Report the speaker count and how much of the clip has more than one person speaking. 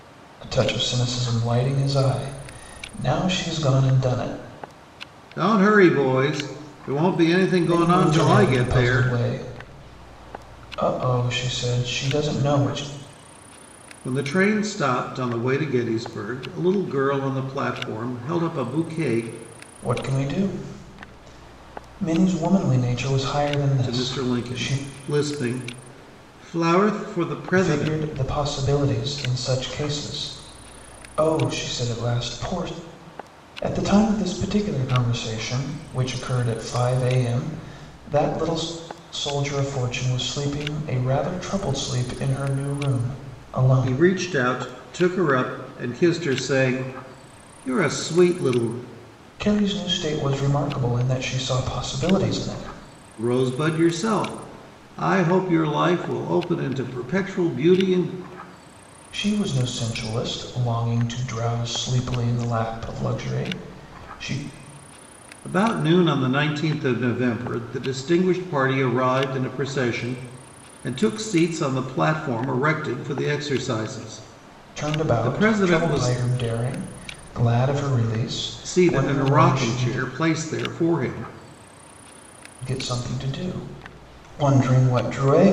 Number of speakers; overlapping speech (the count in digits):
2, about 7%